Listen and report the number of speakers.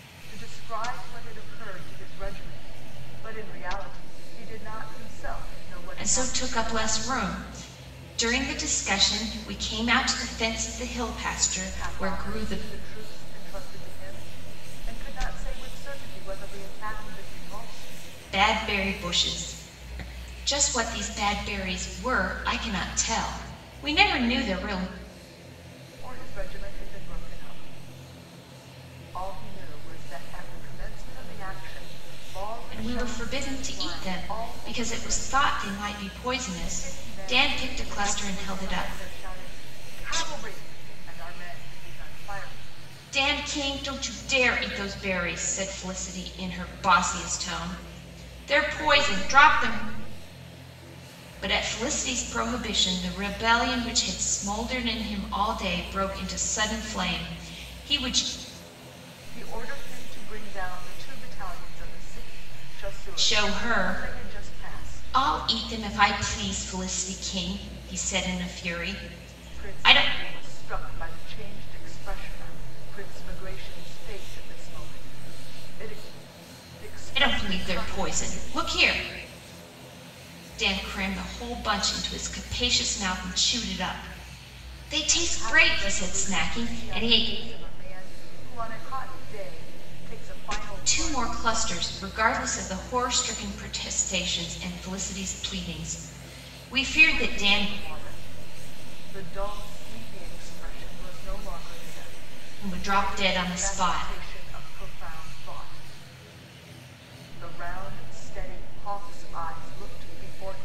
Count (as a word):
two